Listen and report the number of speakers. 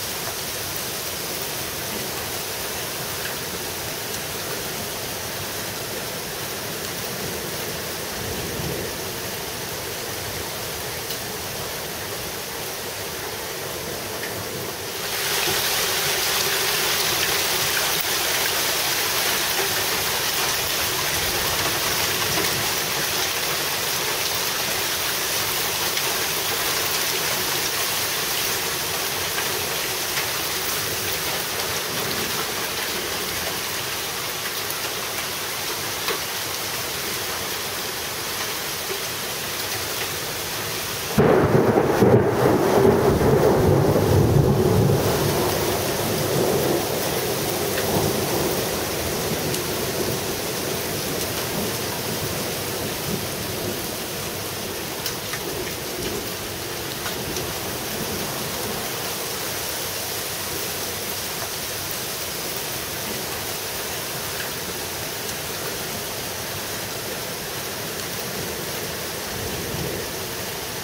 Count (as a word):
zero